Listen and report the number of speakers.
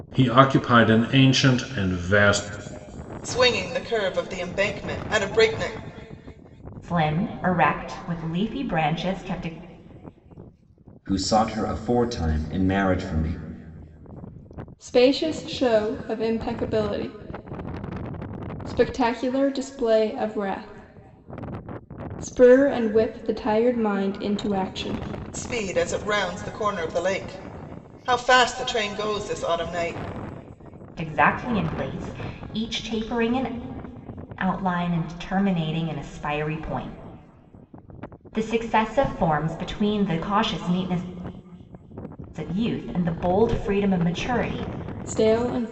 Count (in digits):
5